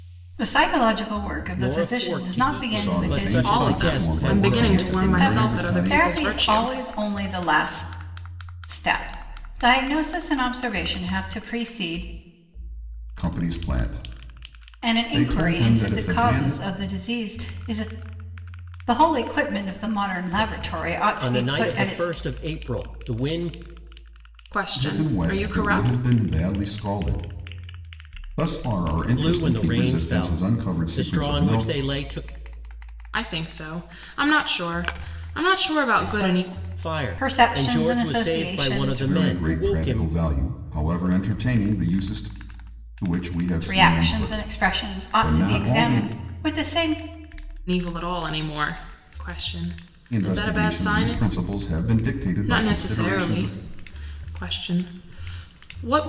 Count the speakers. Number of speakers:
4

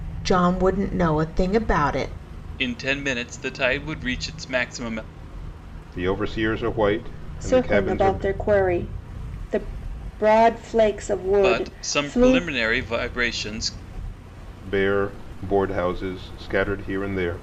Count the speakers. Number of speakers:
4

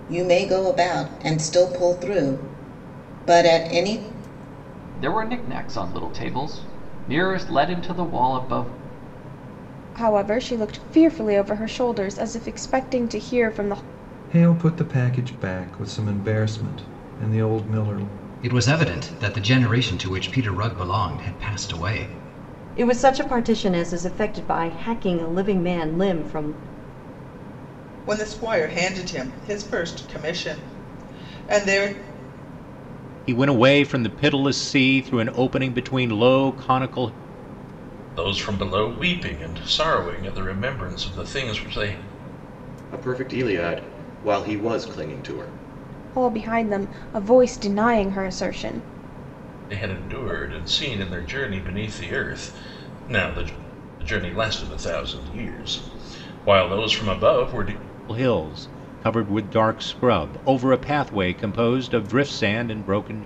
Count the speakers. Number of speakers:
10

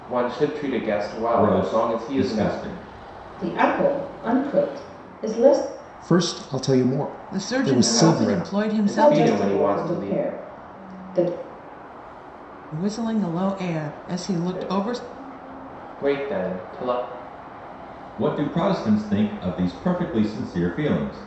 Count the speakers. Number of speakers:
5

